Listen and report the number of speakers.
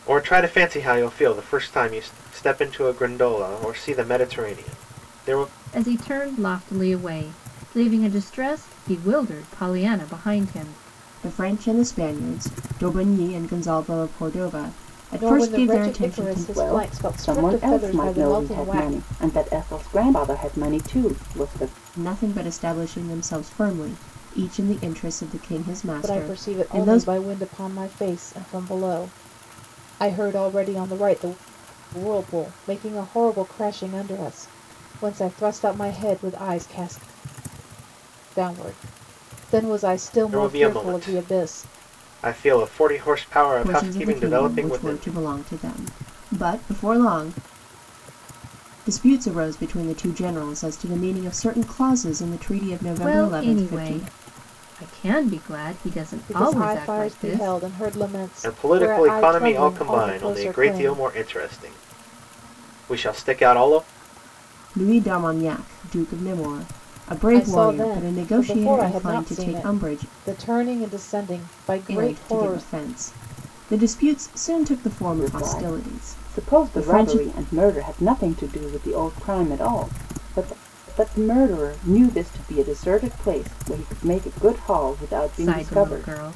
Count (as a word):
five